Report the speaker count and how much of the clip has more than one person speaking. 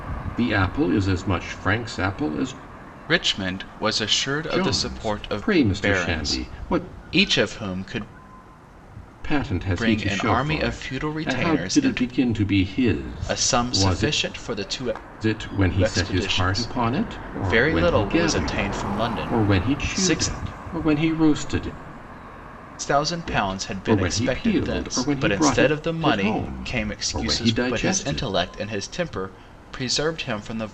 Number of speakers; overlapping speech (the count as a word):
two, about 47%